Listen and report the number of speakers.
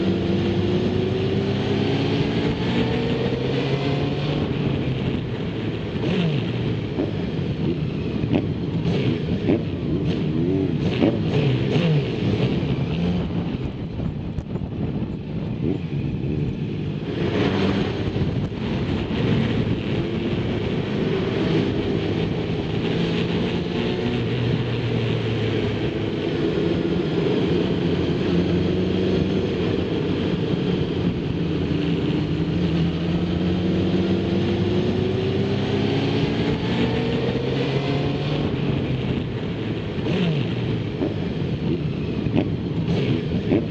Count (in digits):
0